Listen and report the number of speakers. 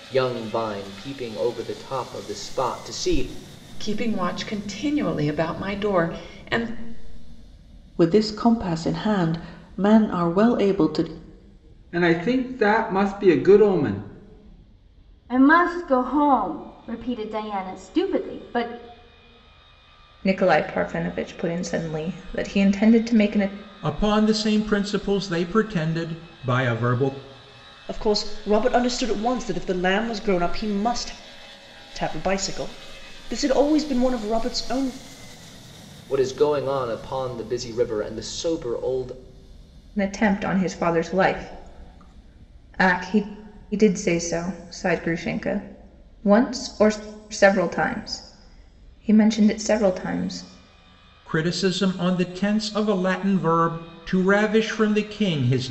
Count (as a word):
eight